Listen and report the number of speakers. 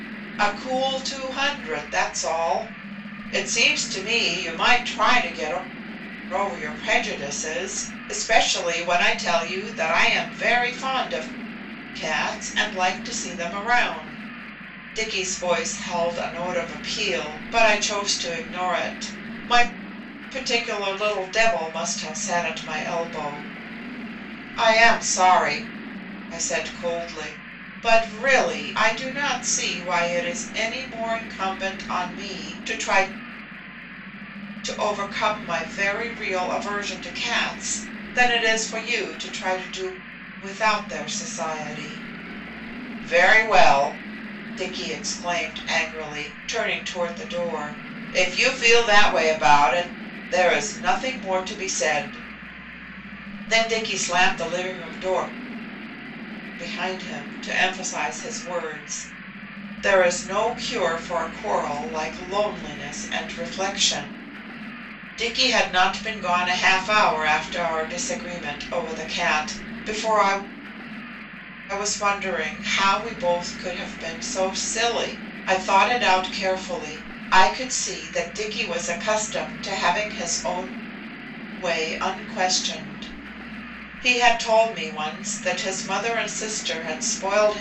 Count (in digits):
1